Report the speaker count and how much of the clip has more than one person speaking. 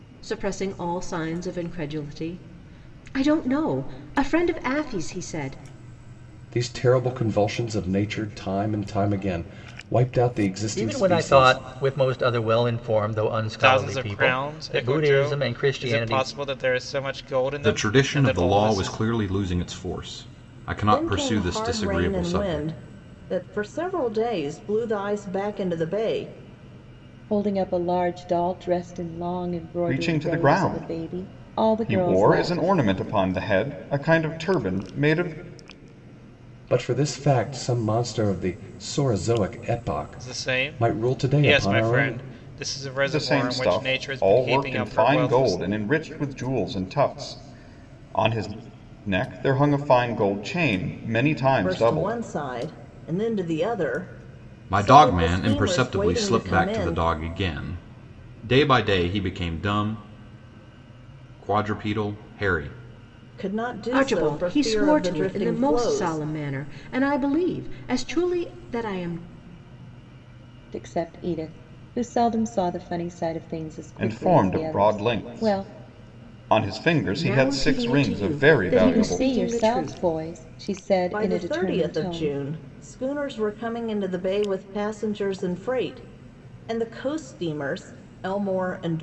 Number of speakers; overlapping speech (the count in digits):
8, about 29%